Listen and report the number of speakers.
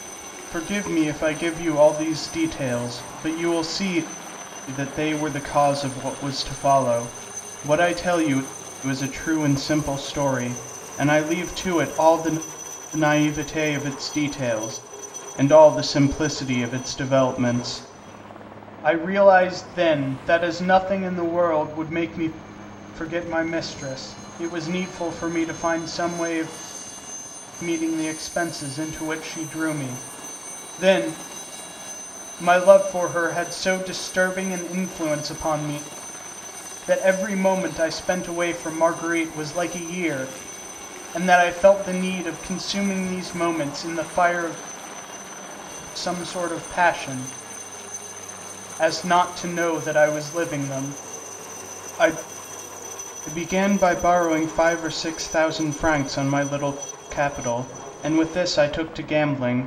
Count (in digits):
1